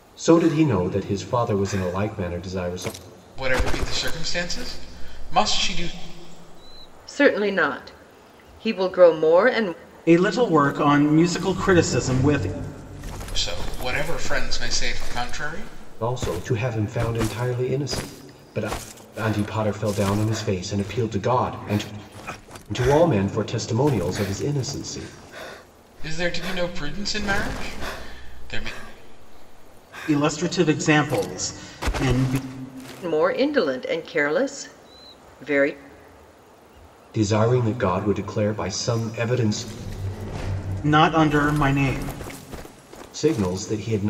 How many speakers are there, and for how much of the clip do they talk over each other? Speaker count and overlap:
four, no overlap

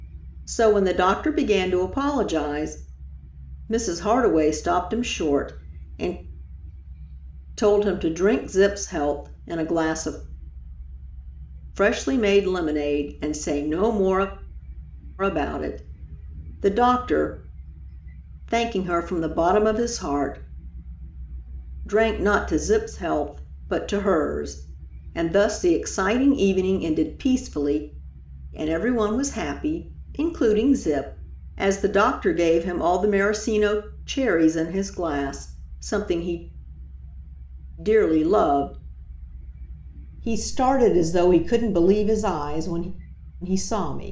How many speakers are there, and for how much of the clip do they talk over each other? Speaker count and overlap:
one, no overlap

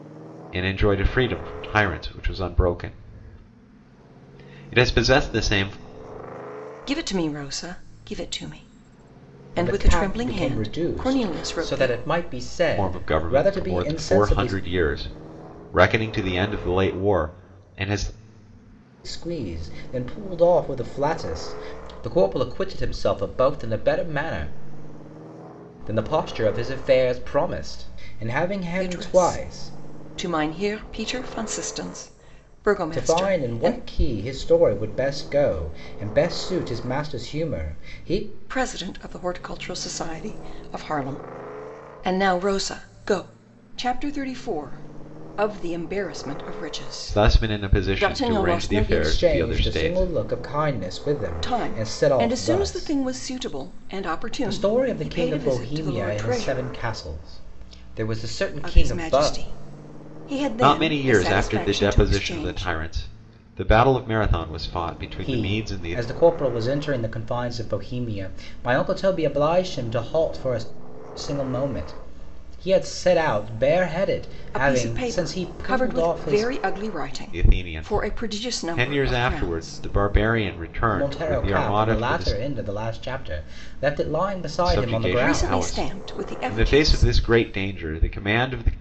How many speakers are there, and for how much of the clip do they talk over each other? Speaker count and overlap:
three, about 28%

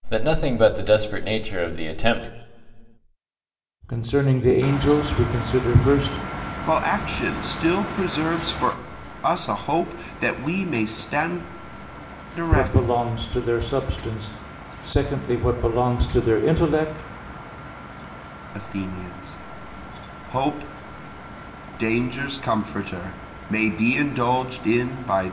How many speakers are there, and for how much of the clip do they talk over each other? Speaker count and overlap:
three, about 2%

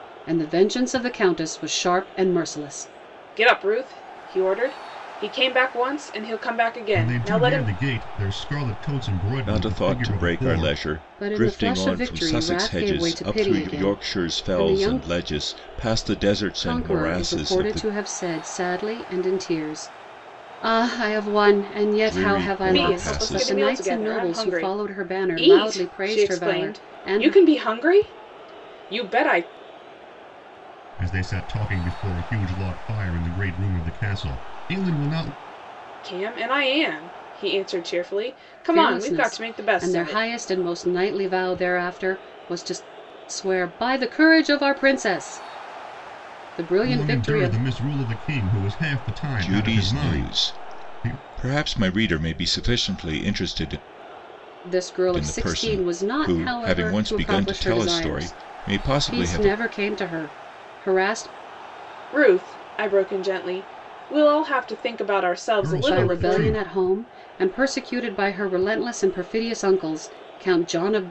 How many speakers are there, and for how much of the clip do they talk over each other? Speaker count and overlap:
four, about 31%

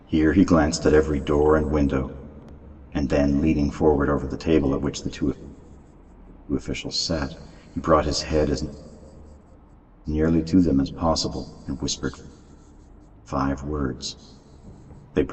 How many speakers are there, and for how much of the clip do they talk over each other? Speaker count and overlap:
one, no overlap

